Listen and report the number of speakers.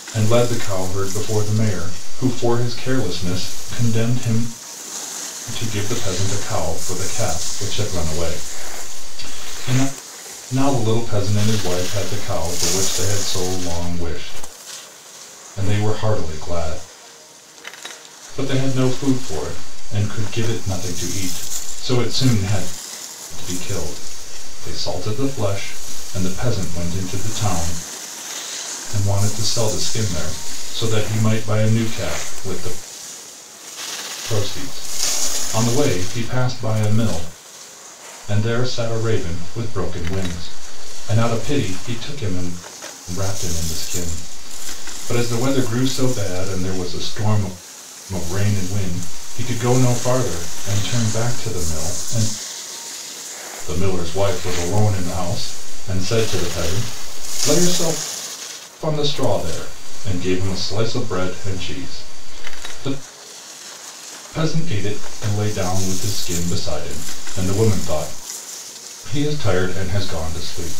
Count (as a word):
one